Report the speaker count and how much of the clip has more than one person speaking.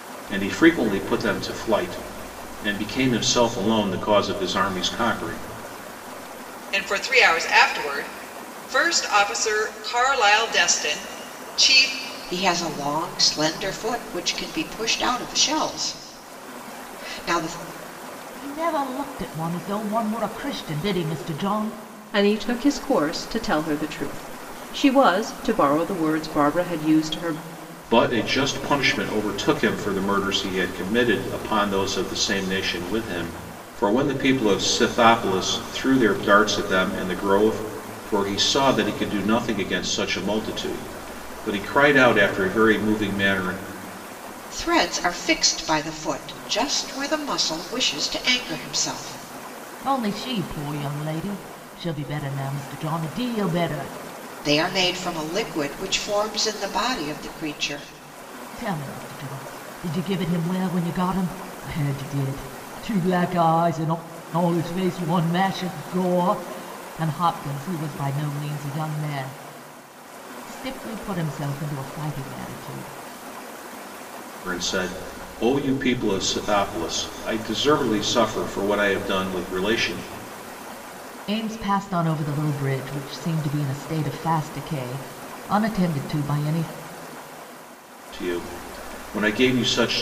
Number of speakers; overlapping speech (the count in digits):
5, no overlap